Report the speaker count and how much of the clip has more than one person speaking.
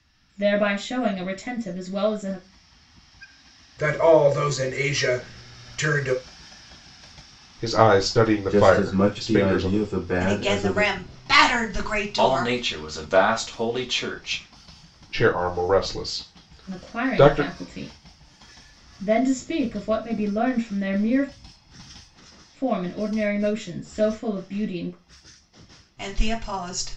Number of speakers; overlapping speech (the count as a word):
six, about 13%